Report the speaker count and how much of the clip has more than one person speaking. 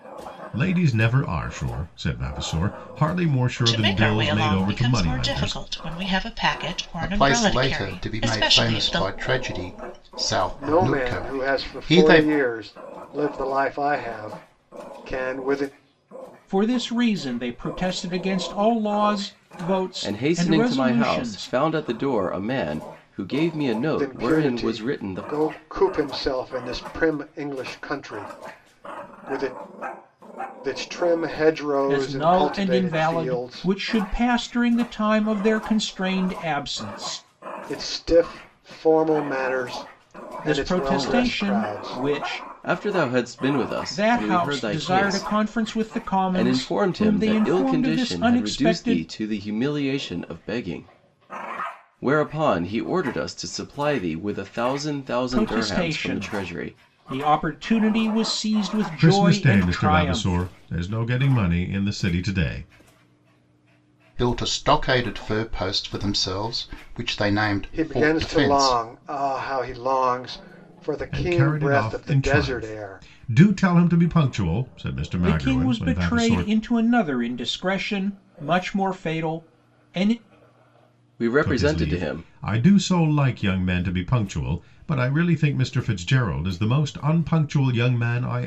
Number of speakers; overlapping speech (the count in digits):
6, about 29%